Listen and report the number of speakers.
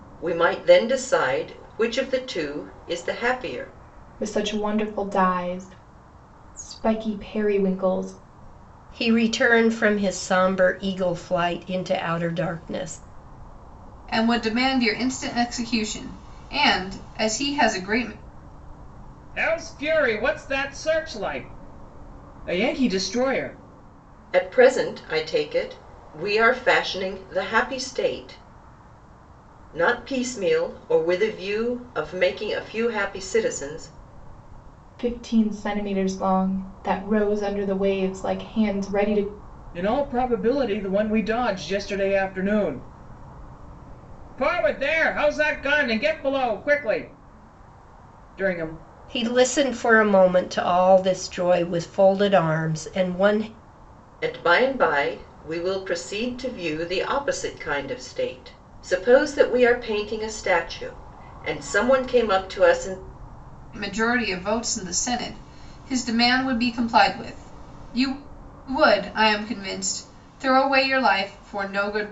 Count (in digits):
5